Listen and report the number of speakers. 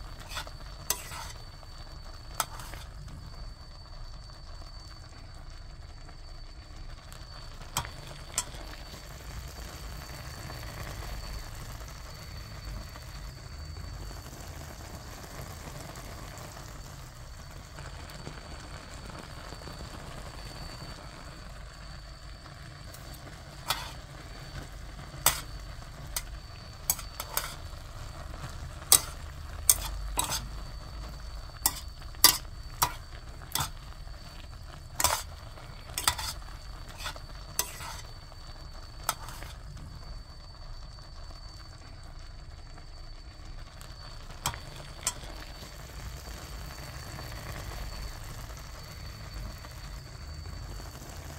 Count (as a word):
zero